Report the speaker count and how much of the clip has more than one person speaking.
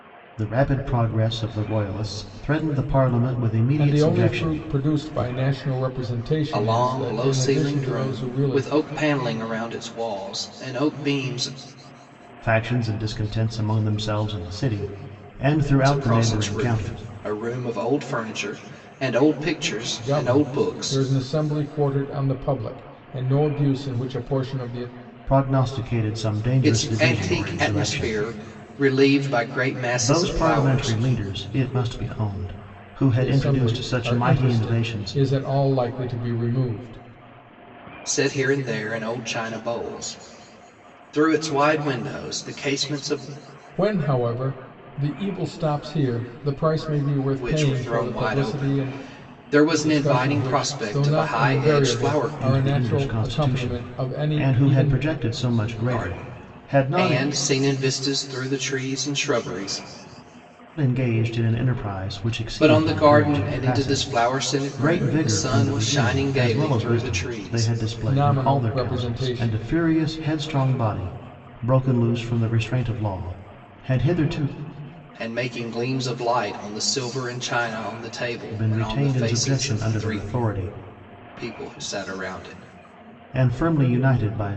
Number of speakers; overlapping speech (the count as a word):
three, about 32%